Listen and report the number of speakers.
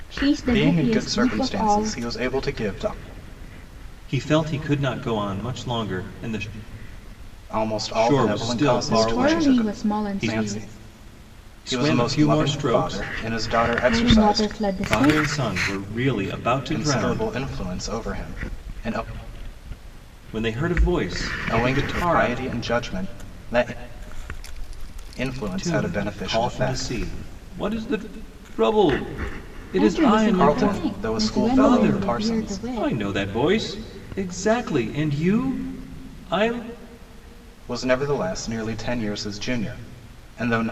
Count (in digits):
3